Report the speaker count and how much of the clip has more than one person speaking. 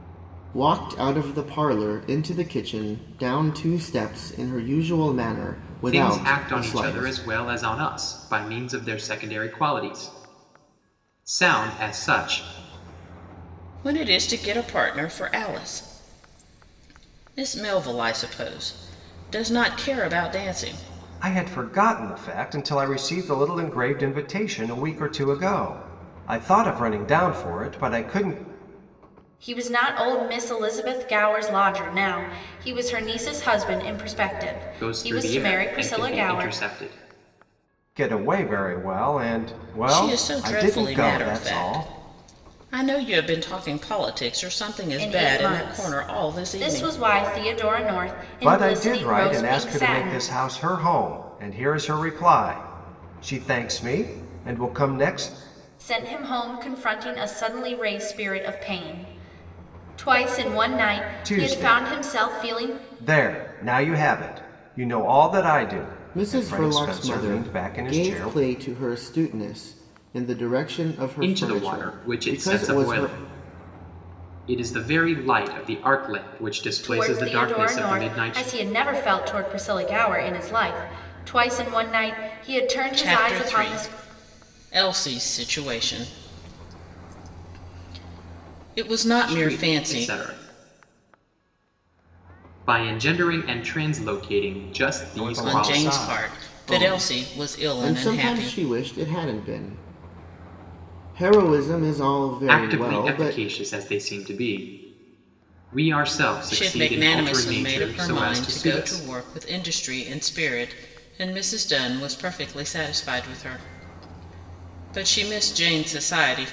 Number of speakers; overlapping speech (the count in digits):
5, about 22%